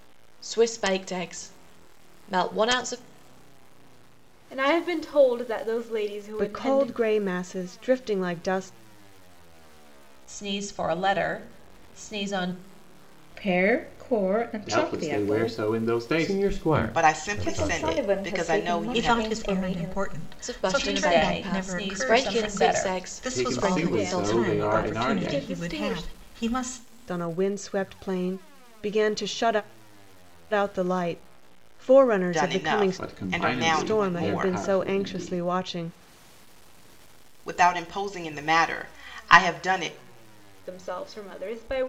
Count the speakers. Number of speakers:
10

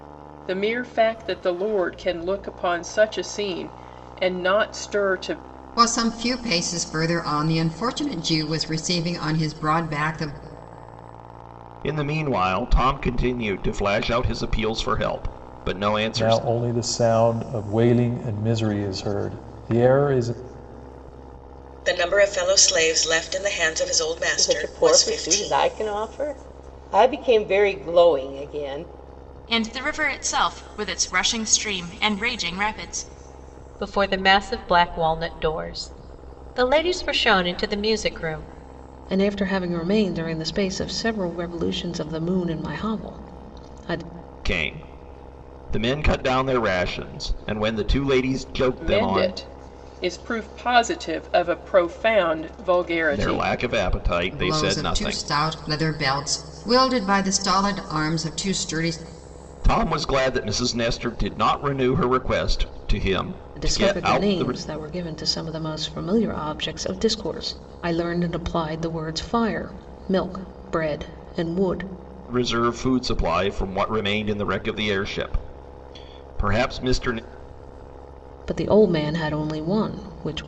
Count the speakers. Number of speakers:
9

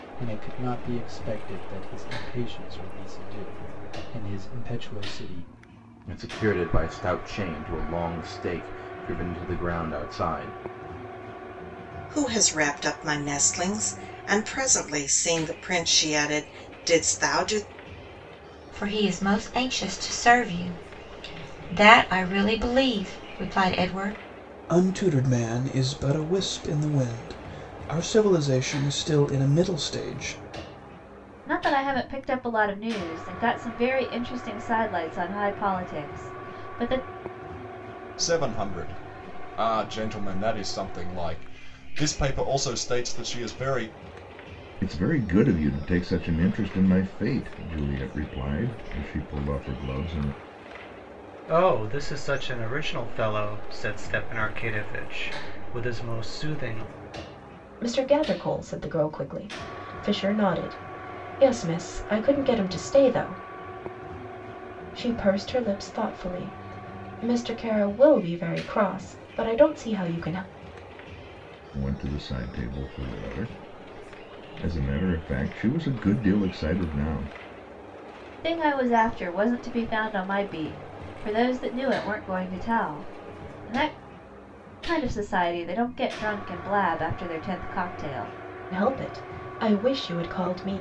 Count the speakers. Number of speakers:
10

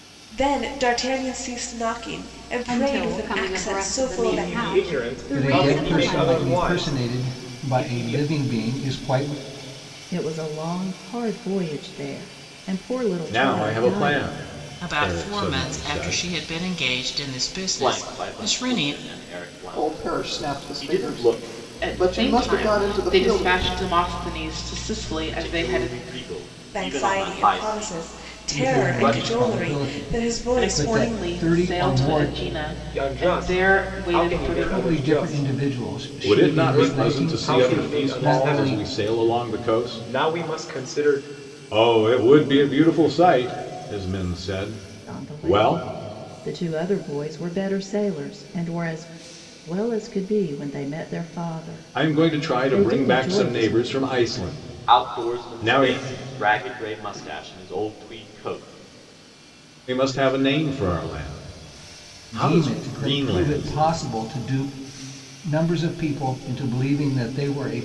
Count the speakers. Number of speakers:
10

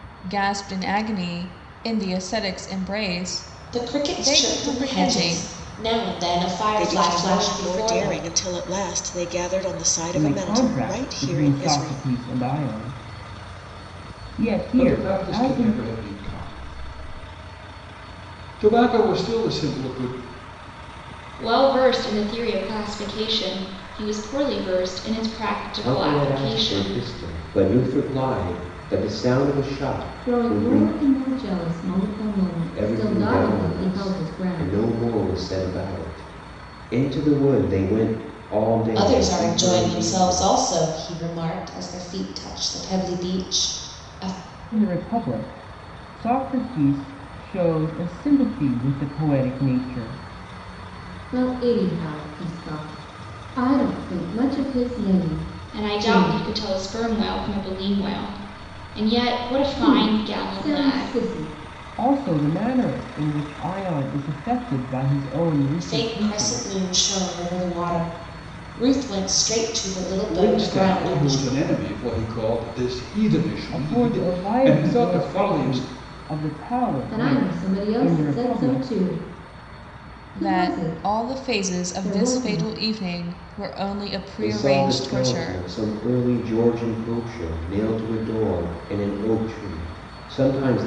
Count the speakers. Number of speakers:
8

